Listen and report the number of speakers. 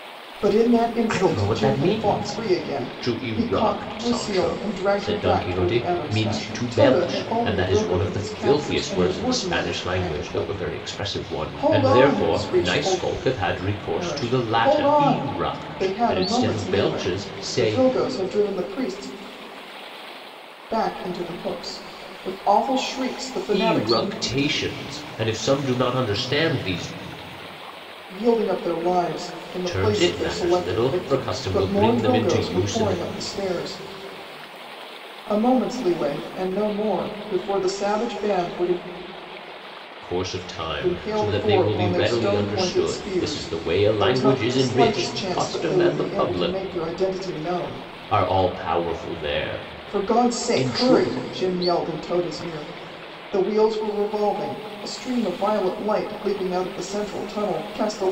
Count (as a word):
two